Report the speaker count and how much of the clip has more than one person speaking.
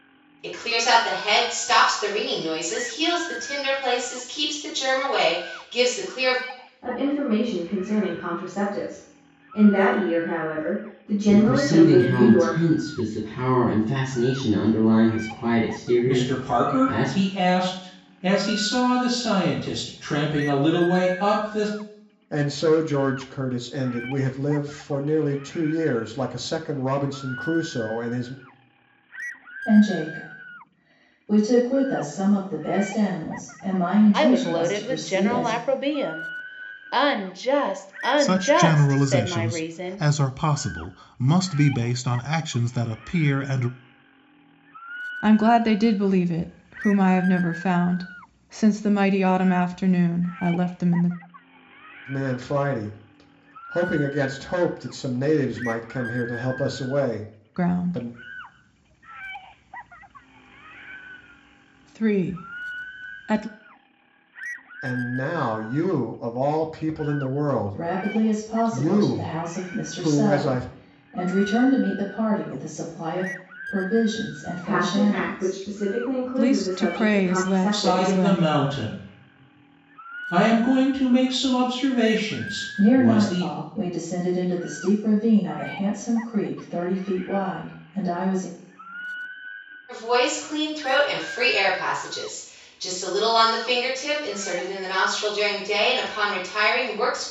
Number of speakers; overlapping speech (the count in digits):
9, about 14%